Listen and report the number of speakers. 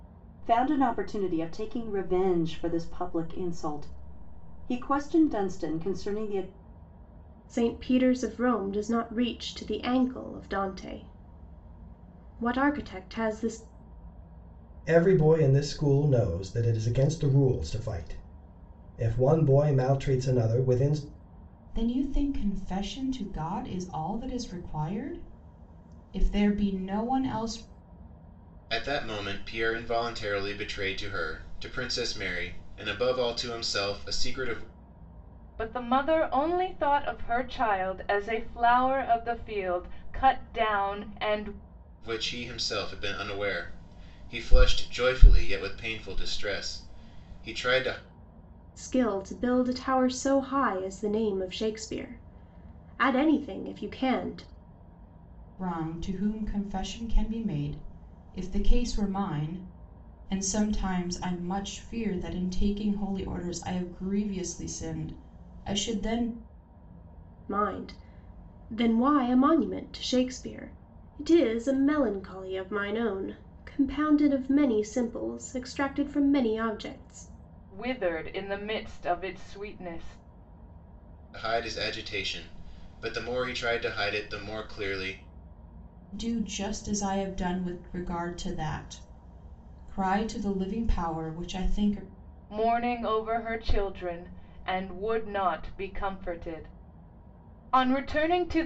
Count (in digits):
6